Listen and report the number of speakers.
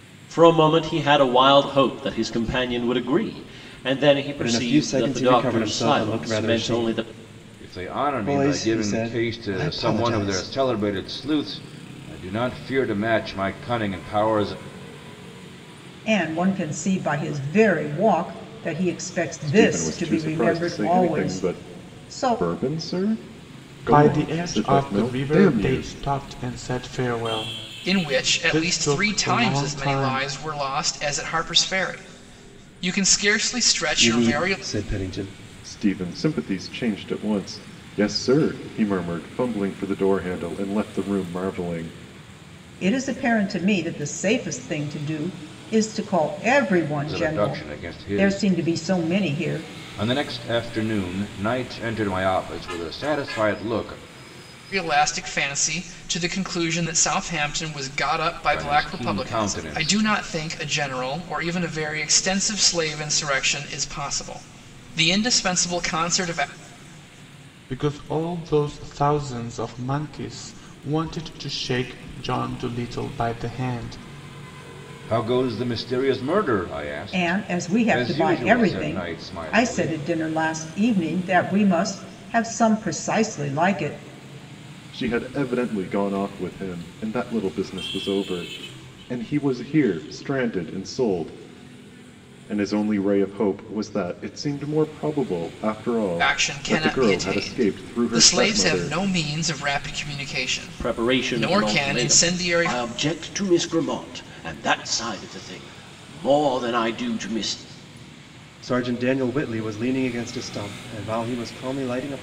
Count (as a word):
seven